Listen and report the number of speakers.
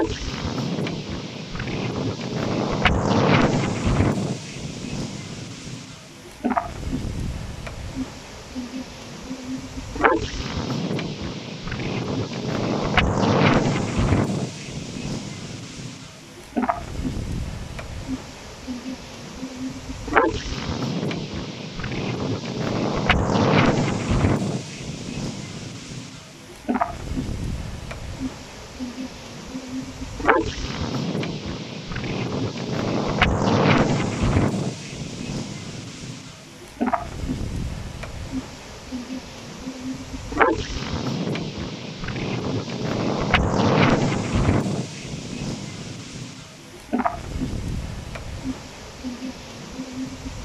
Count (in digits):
0